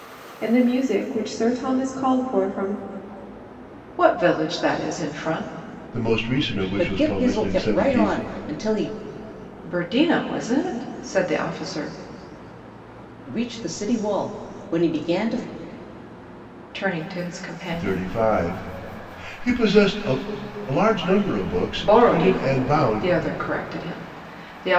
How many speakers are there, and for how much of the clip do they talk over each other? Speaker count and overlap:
4, about 12%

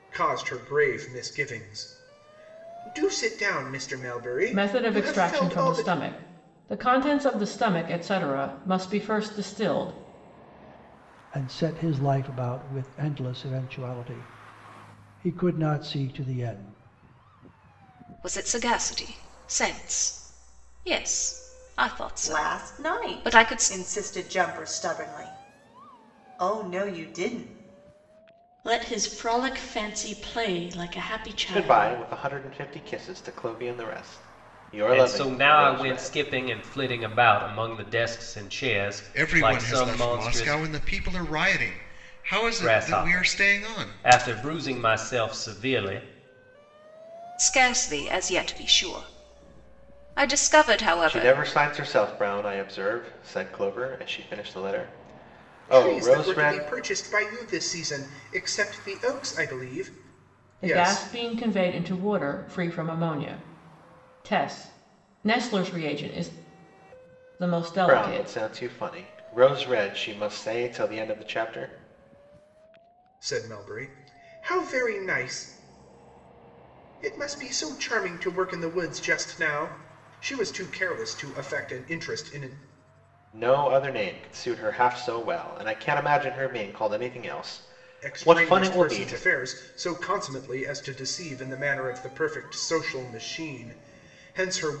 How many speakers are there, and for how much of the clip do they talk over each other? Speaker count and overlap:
9, about 12%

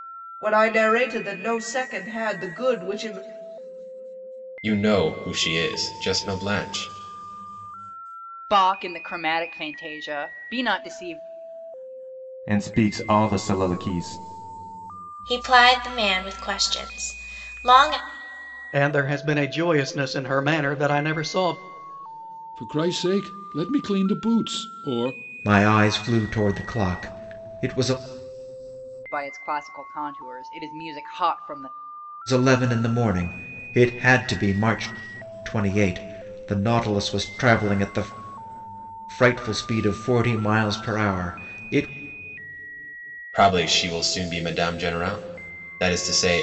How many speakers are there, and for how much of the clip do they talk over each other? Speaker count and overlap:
8, no overlap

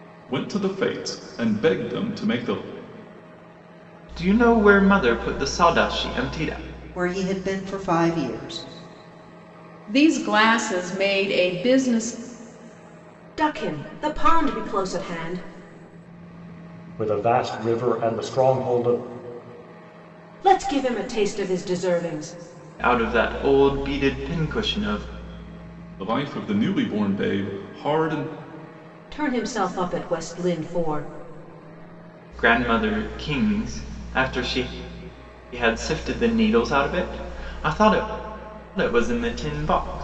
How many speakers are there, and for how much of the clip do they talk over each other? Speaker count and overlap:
6, no overlap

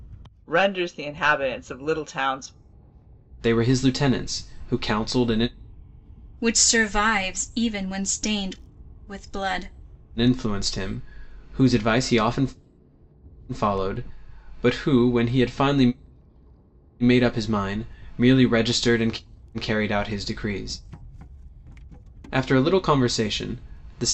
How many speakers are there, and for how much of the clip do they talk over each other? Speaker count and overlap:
3, no overlap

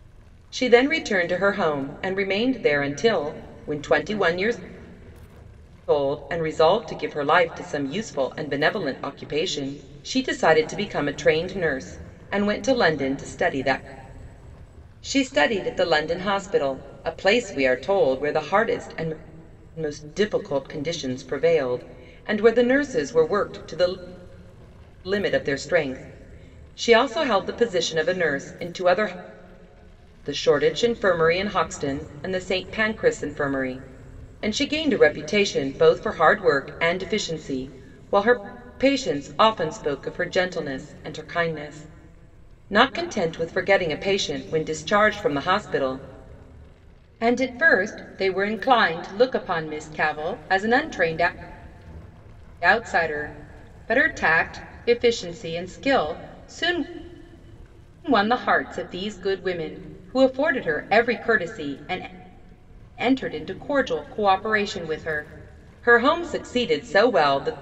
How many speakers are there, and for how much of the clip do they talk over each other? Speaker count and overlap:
1, no overlap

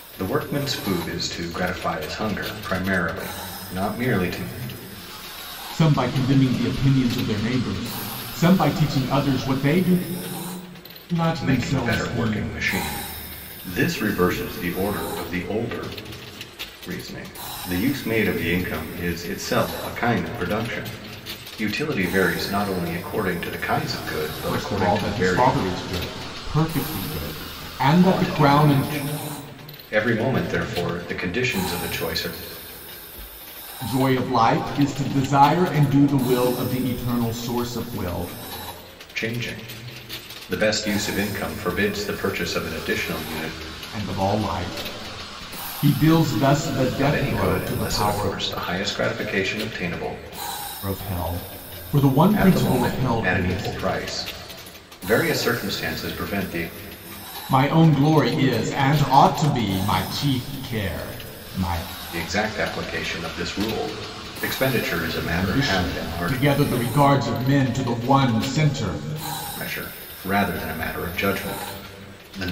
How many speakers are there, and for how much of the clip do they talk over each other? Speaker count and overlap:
2, about 10%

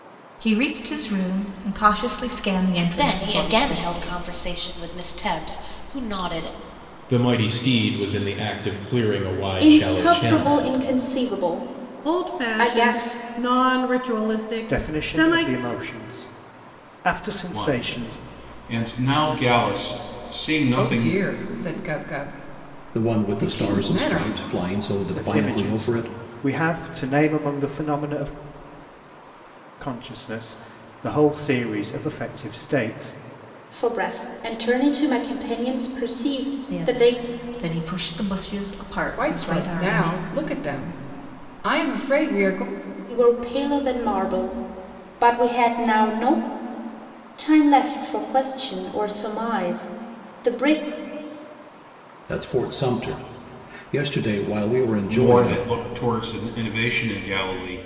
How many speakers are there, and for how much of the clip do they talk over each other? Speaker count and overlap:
9, about 17%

